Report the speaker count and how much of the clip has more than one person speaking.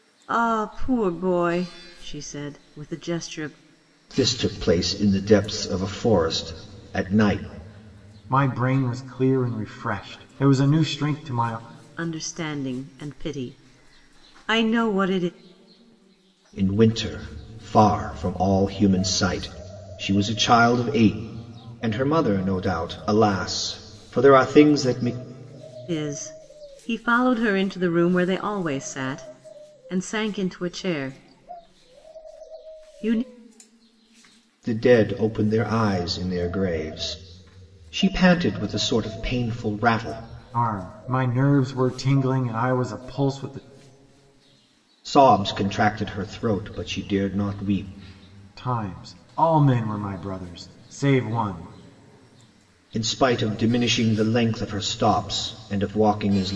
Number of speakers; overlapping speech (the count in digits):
3, no overlap